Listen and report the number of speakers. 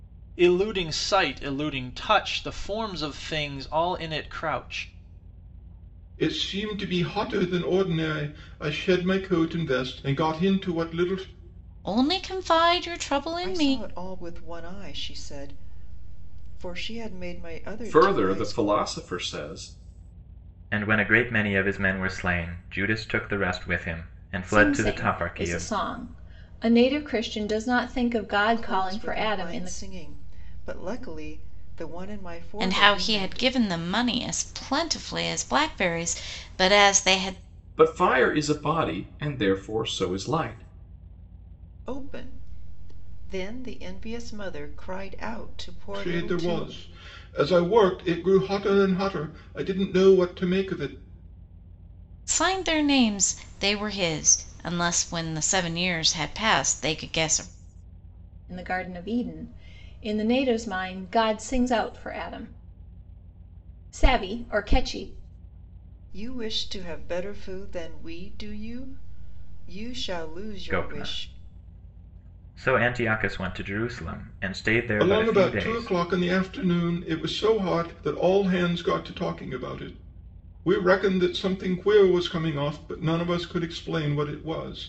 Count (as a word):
seven